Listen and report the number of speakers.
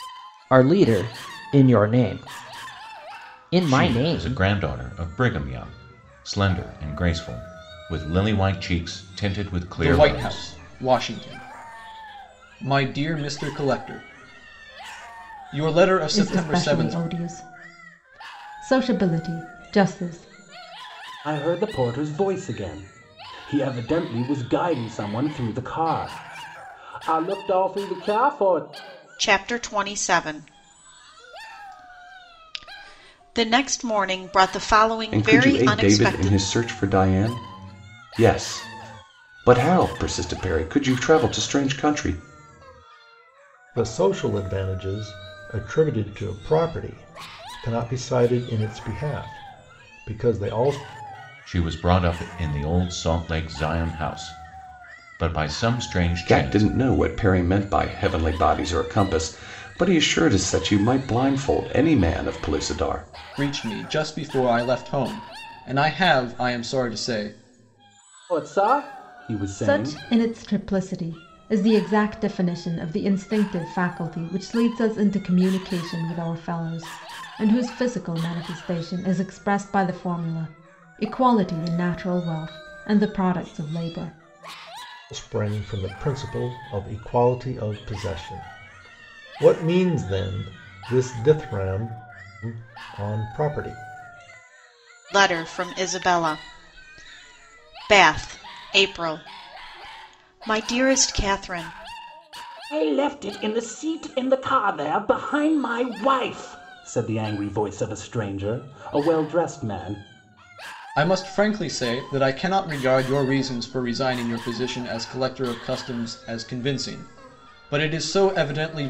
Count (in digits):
8